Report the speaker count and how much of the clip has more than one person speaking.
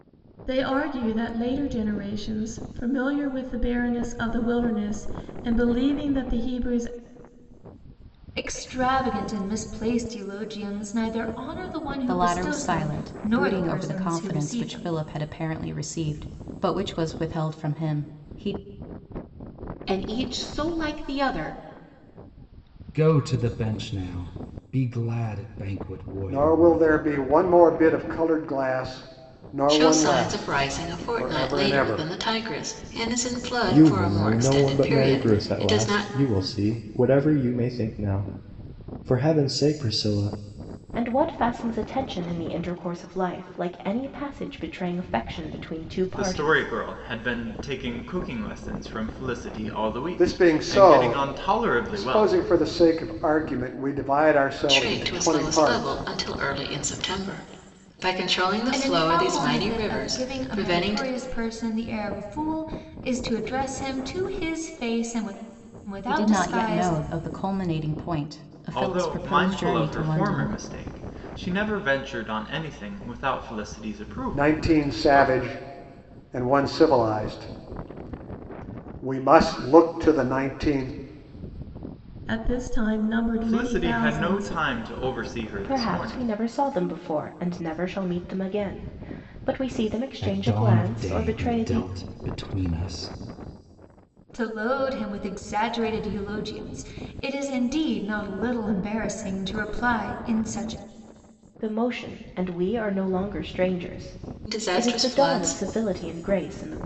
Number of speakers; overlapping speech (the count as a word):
ten, about 22%